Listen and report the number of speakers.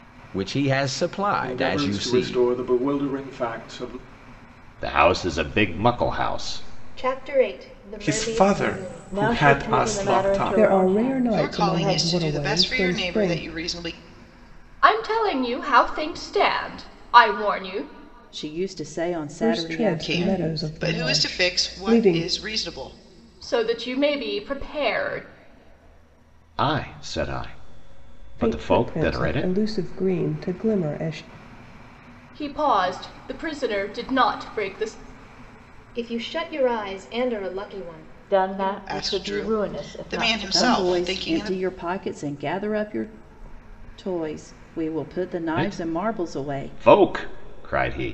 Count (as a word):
ten